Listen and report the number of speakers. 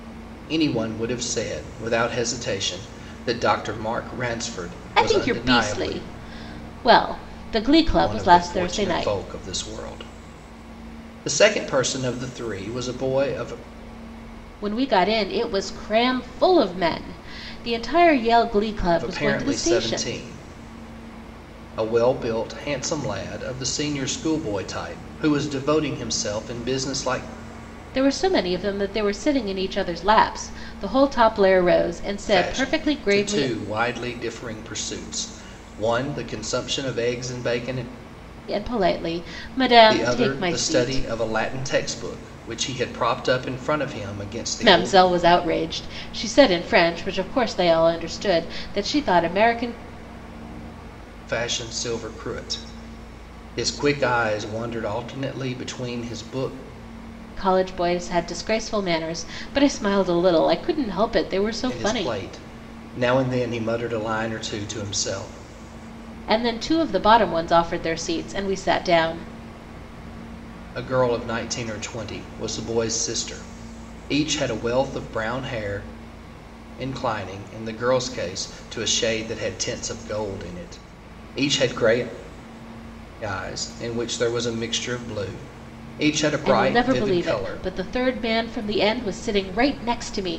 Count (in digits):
2